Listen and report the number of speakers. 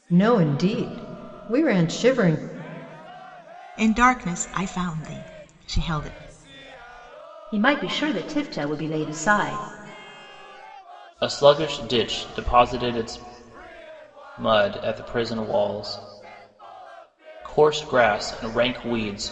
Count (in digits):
4